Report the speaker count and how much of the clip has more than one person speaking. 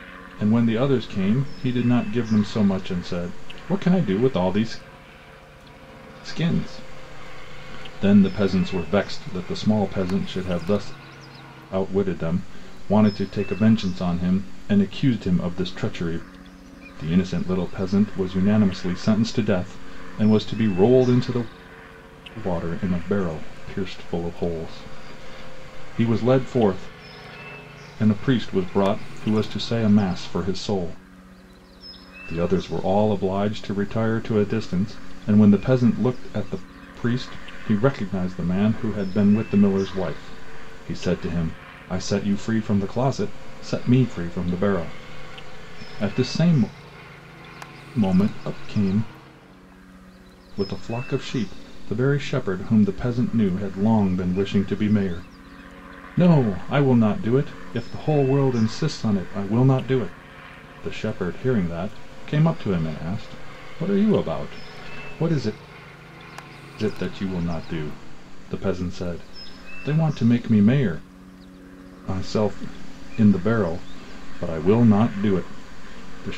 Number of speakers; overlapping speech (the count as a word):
one, no overlap